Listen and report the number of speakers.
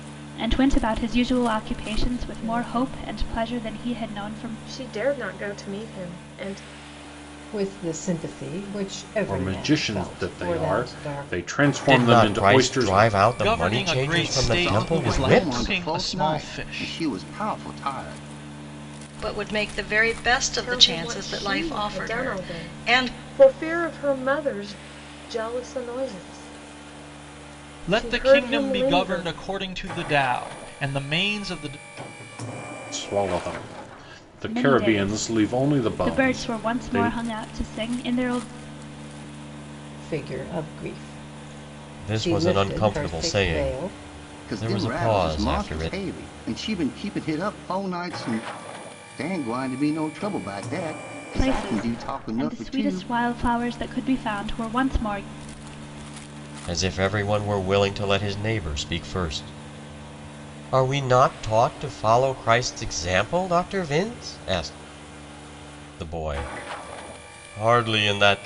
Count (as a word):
eight